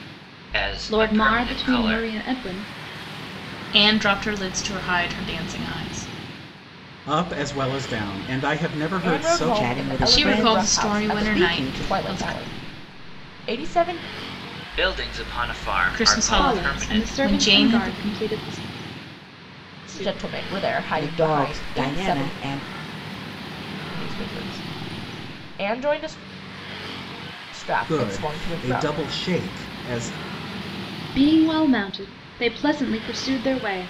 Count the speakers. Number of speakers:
six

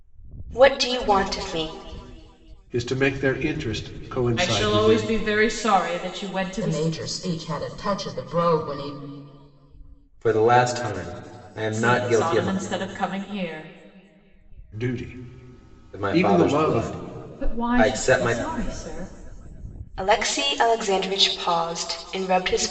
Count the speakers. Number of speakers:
five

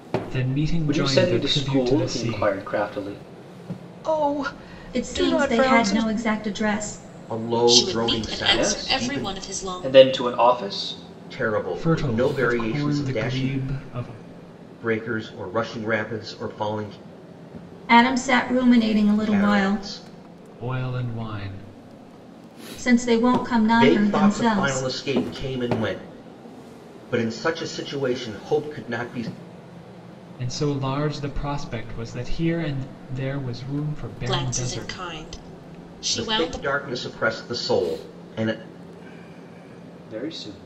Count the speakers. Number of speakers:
six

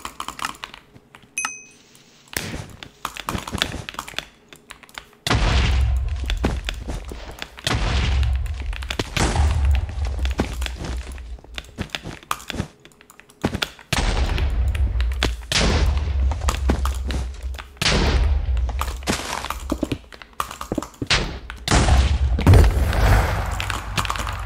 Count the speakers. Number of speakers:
zero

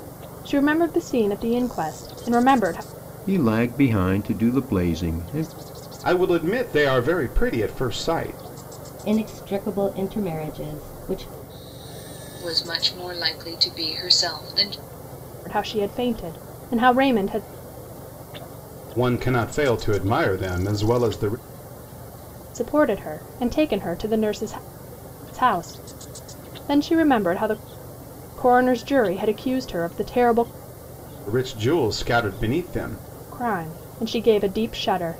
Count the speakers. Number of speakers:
five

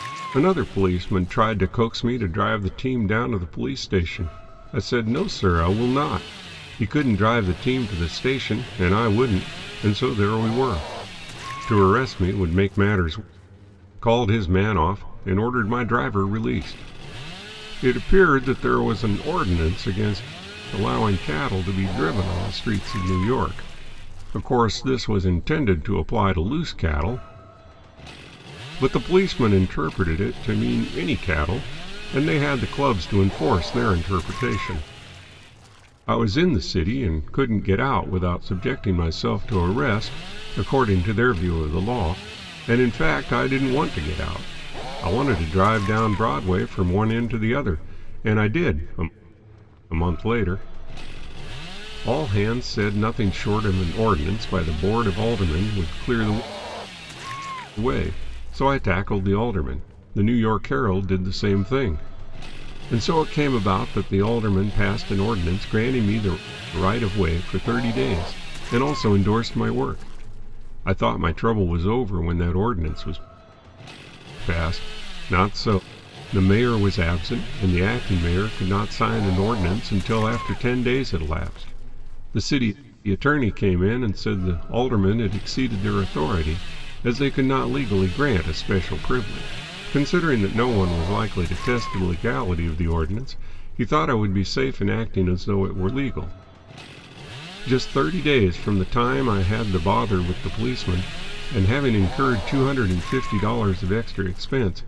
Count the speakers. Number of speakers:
one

